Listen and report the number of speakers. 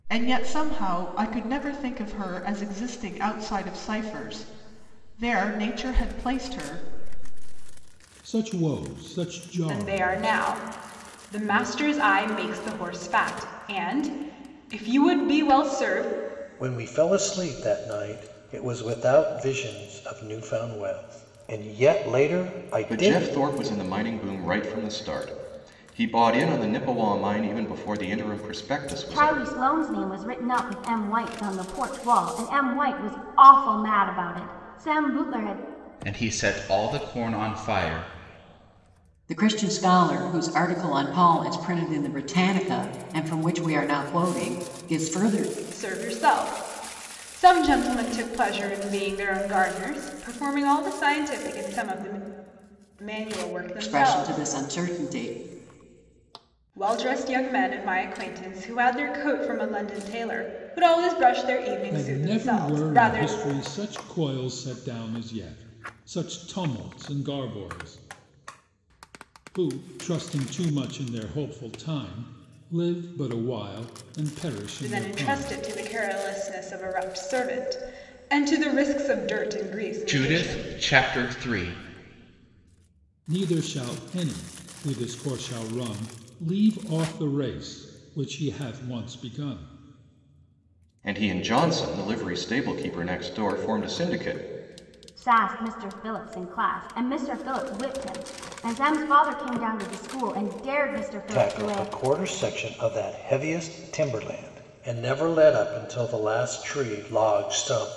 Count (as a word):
eight